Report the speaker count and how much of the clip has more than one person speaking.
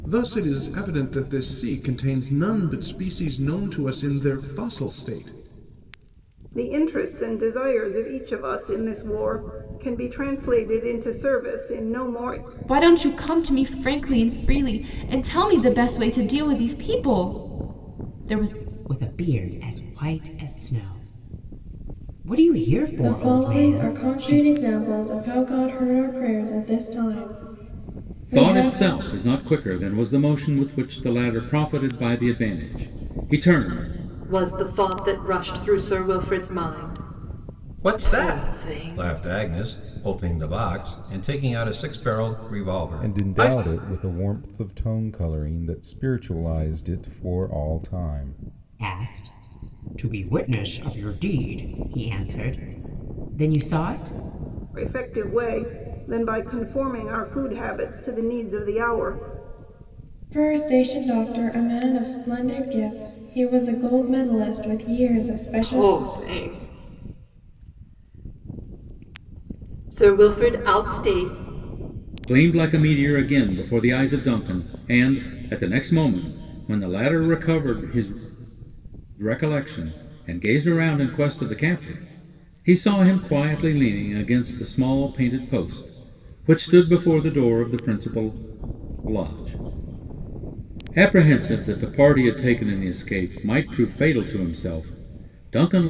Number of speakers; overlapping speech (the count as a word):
nine, about 5%